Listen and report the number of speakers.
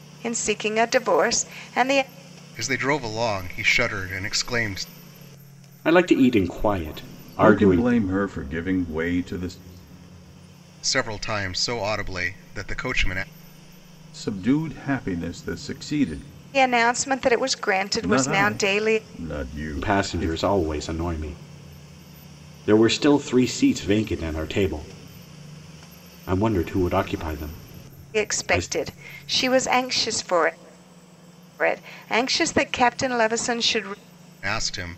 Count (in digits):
4